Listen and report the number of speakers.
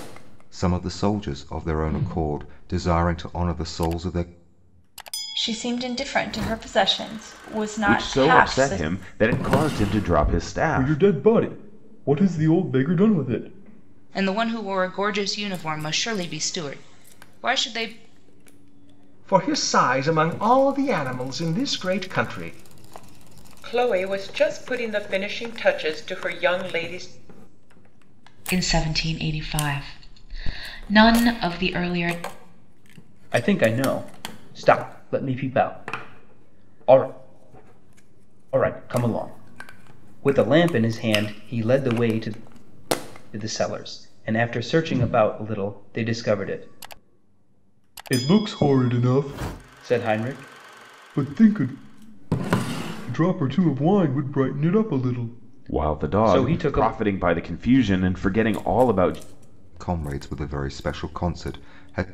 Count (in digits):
8